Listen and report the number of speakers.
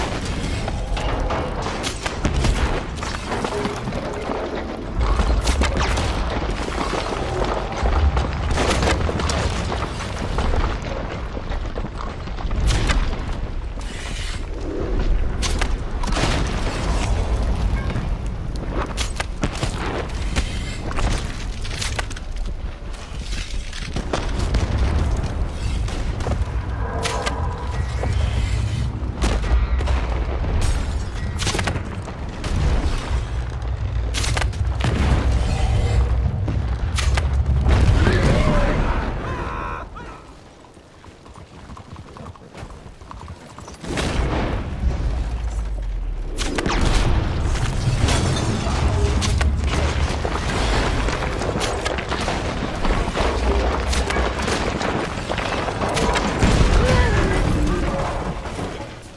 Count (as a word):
zero